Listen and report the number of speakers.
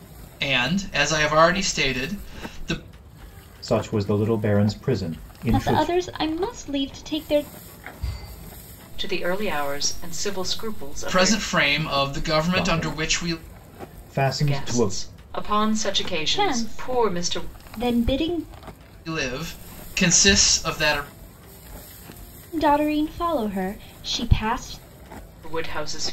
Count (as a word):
four